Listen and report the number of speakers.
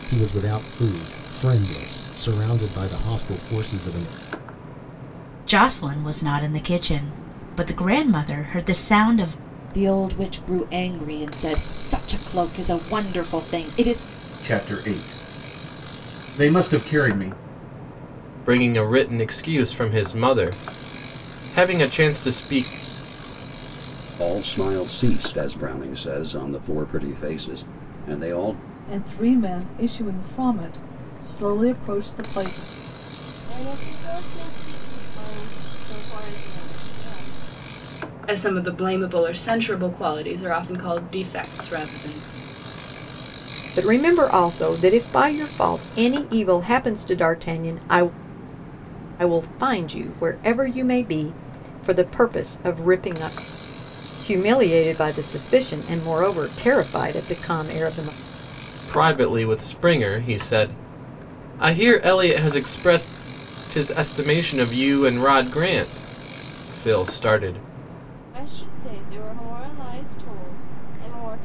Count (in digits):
10